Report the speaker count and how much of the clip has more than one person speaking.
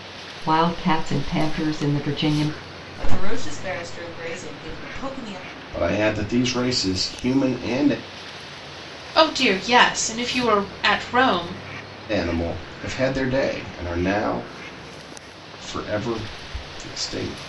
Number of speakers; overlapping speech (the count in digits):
4, no overlap